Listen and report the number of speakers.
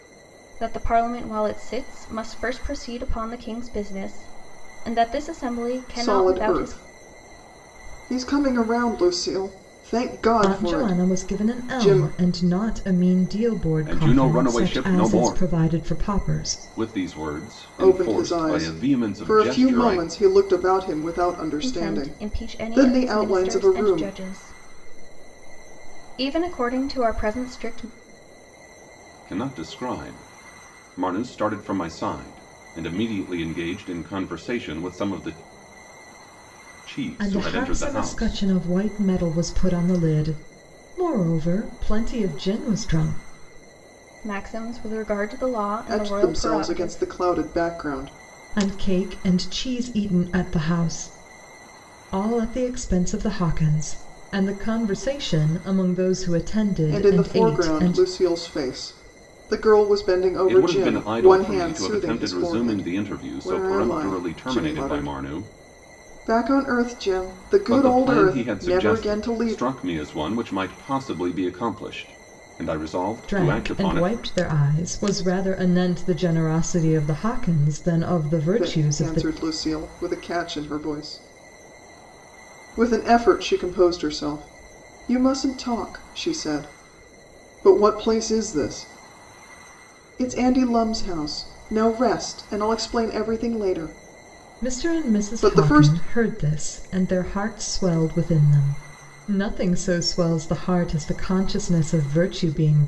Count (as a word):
four